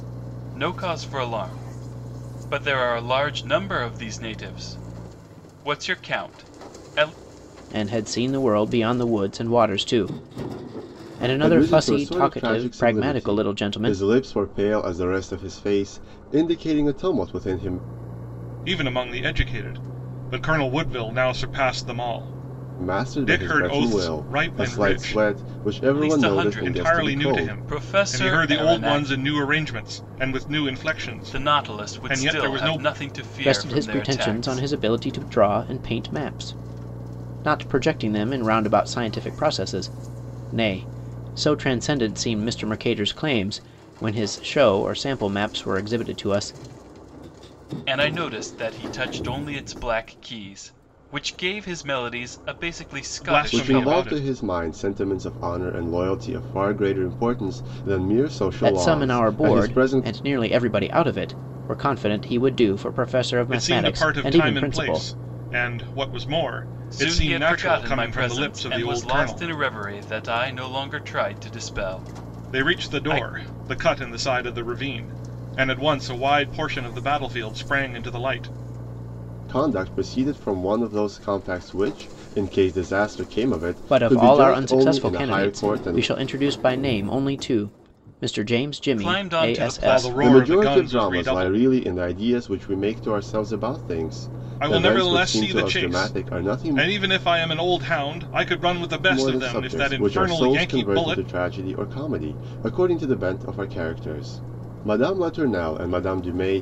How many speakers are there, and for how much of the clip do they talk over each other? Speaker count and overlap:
4, about 26%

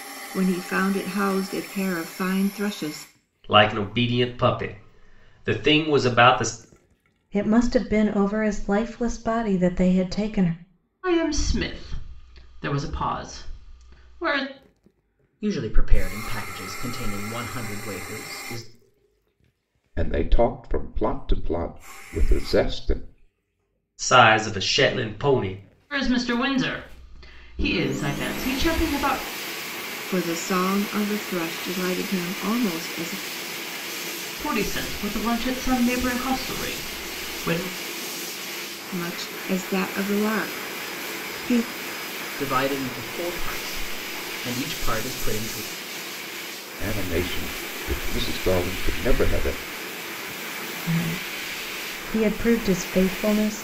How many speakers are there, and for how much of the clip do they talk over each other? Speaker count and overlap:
6, no overlap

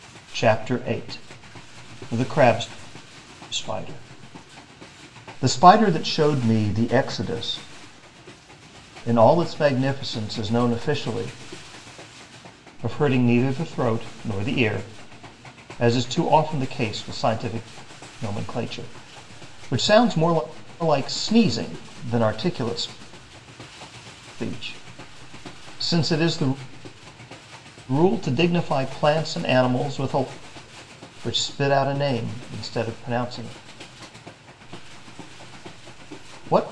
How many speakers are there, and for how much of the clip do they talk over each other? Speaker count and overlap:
1, no overlap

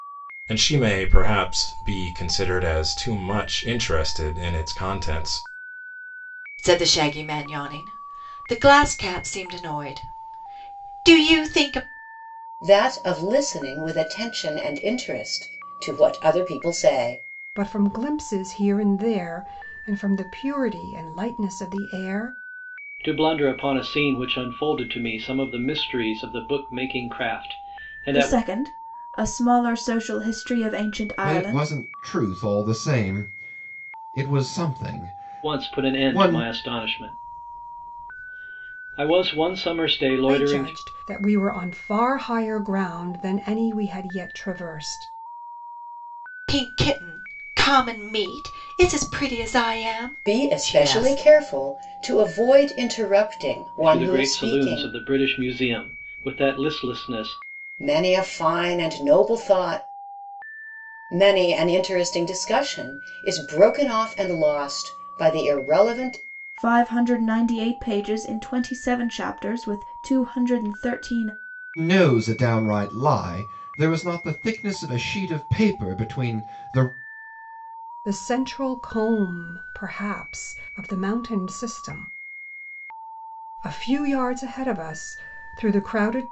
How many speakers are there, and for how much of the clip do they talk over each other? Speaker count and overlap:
7, about 5%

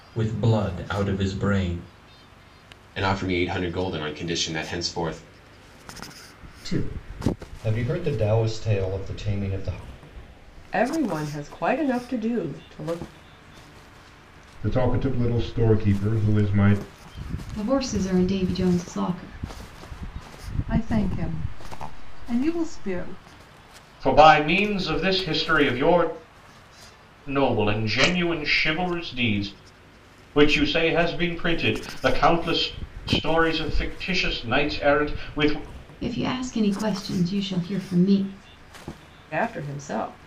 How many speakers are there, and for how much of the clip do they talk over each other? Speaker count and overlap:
9, no overlap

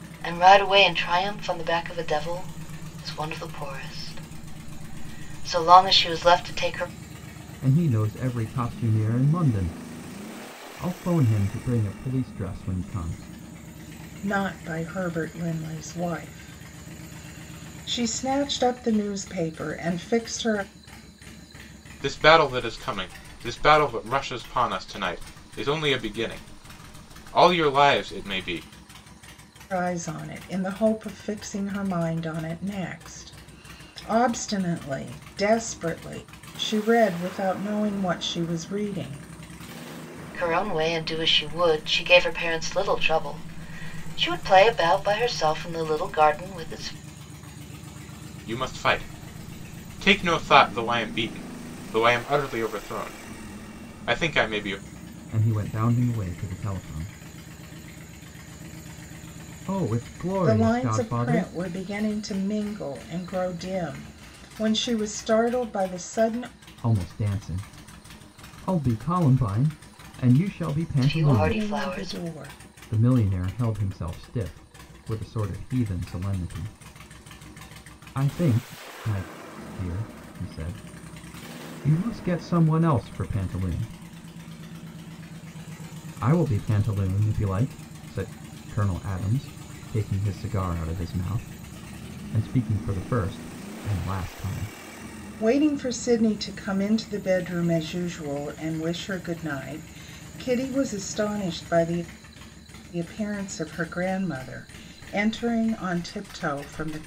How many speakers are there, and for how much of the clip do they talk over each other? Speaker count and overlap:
4, about 2%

